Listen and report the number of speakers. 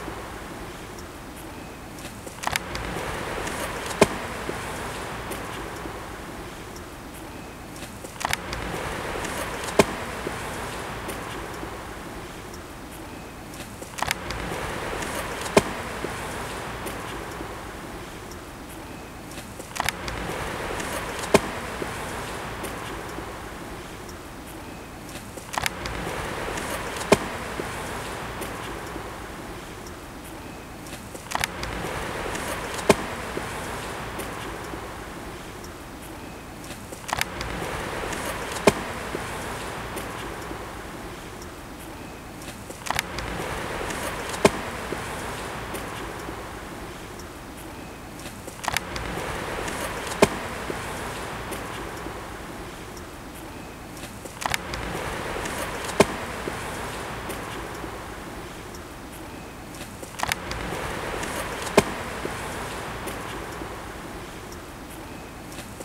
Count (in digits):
0